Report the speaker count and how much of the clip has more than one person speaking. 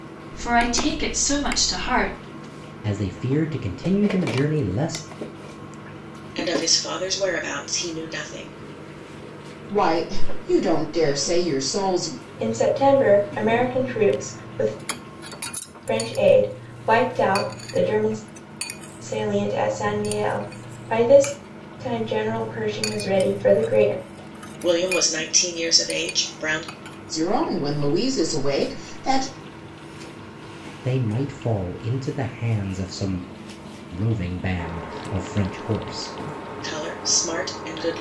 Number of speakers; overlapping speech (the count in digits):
5, no overlap